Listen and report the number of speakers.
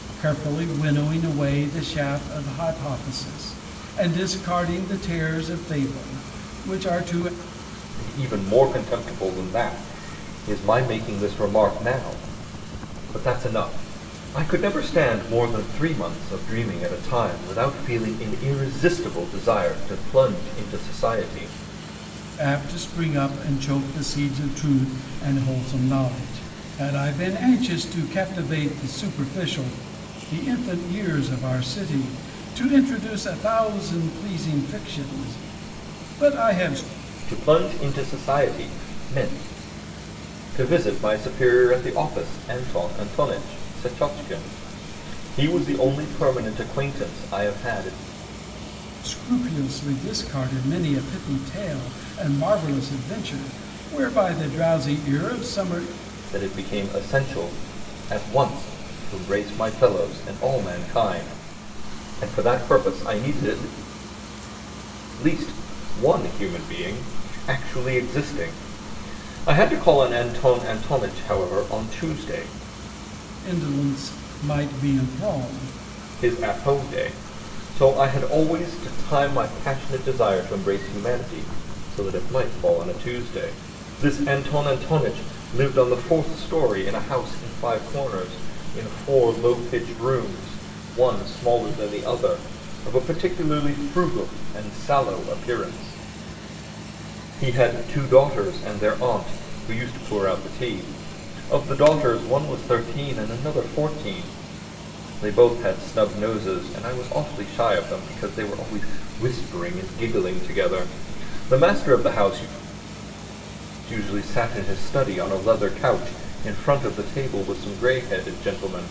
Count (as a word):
two